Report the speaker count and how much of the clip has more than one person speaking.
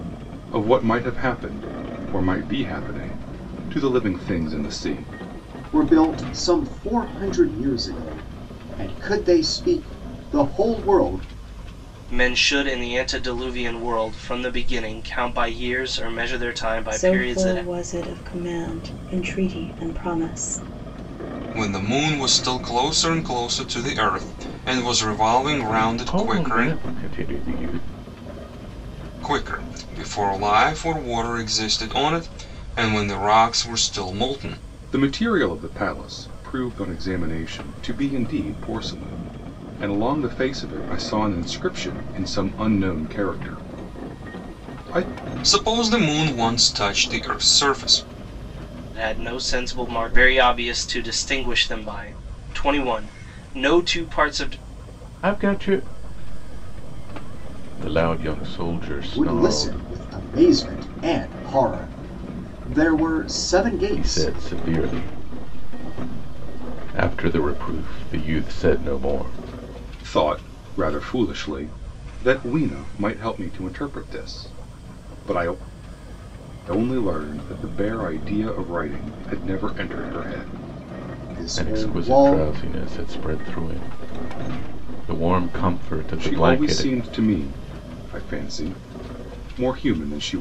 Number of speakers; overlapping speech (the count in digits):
6, about 5%